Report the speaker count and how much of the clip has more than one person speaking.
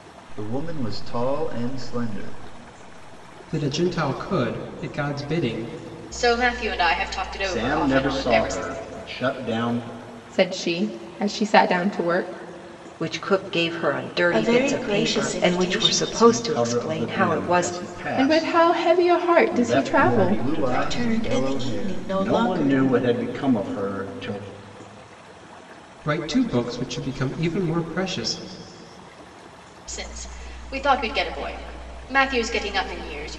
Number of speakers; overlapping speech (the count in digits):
7, about 25%